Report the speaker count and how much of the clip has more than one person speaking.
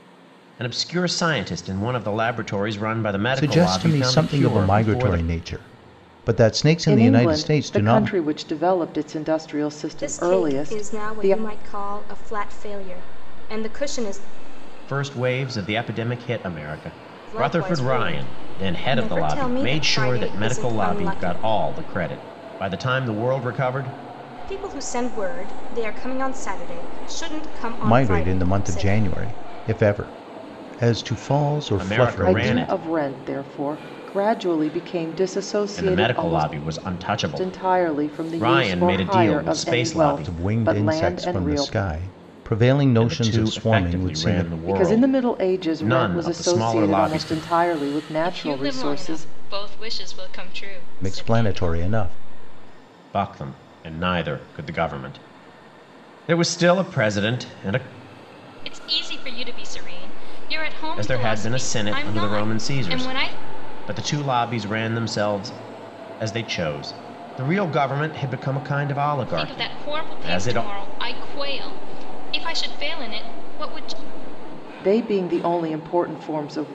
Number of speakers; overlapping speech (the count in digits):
4, about 35%